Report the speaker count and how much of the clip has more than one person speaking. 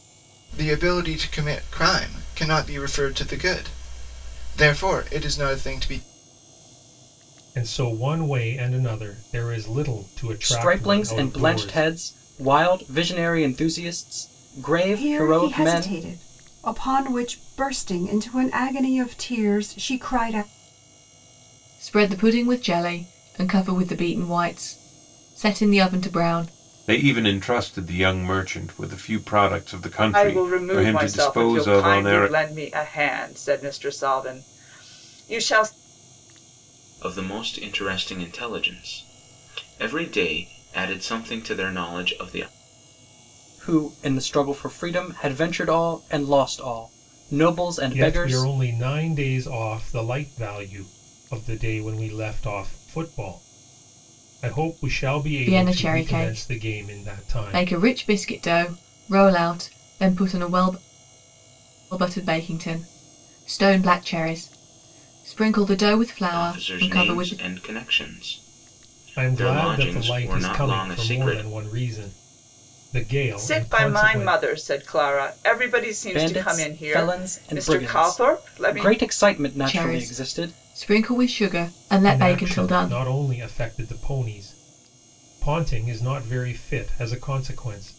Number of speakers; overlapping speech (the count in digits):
8, about 19%